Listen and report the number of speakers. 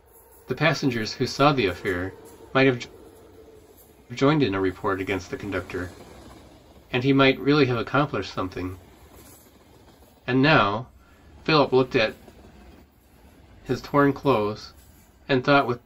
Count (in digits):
1